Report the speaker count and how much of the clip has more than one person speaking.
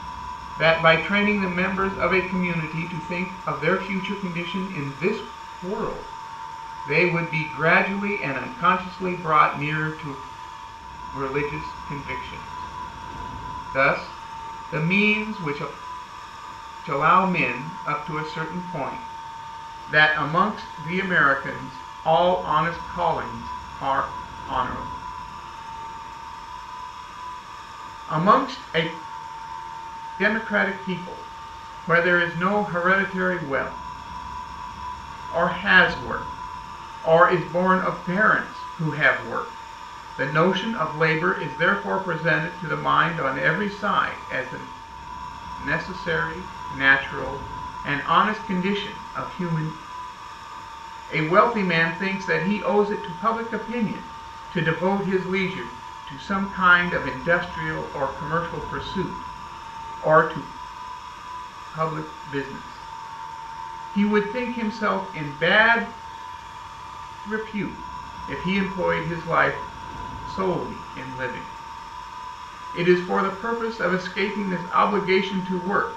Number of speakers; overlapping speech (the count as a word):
one, no overlap